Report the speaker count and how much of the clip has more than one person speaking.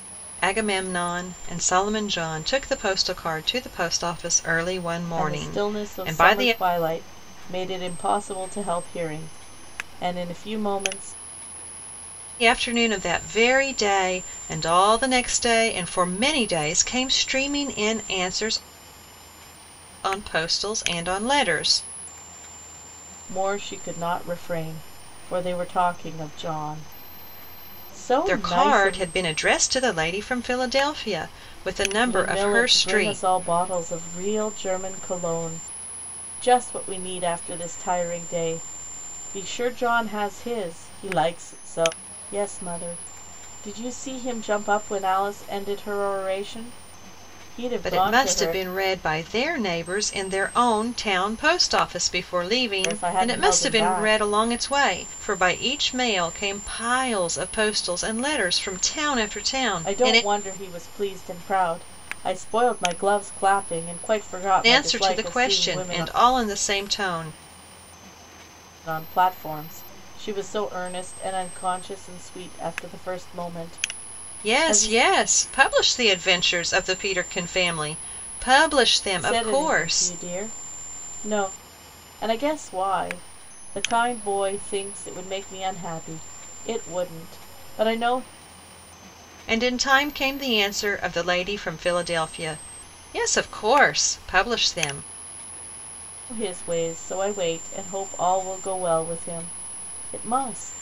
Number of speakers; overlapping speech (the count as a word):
two, about 9%